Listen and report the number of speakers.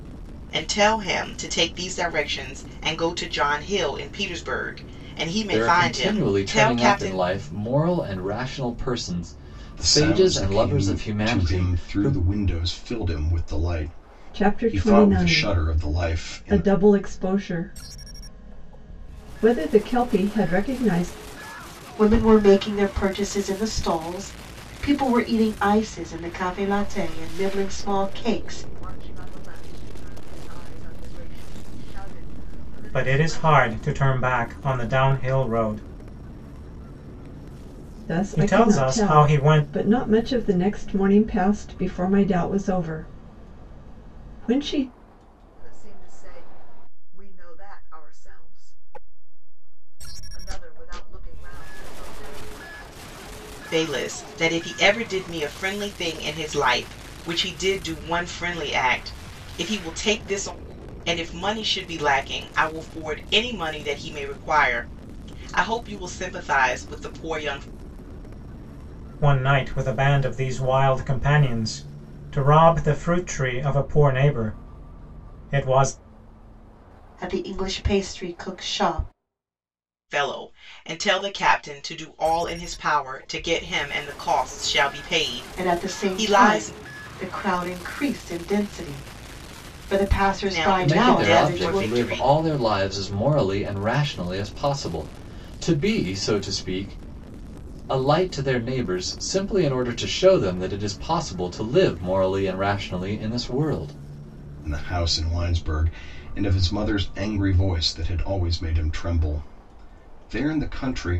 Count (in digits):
7